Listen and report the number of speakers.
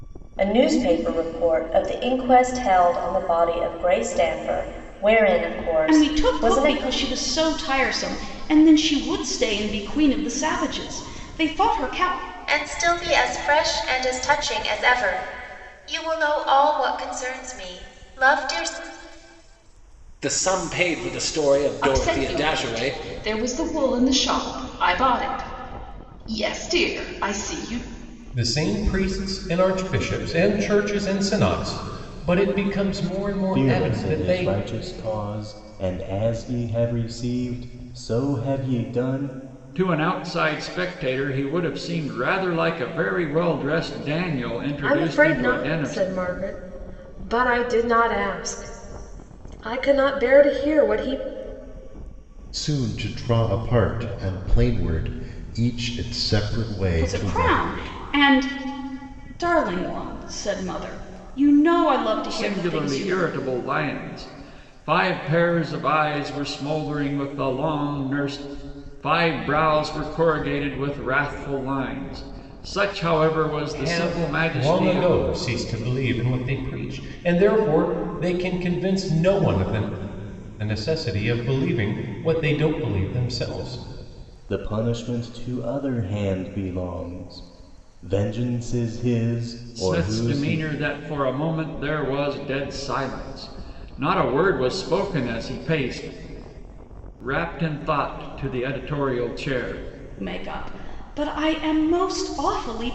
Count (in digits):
10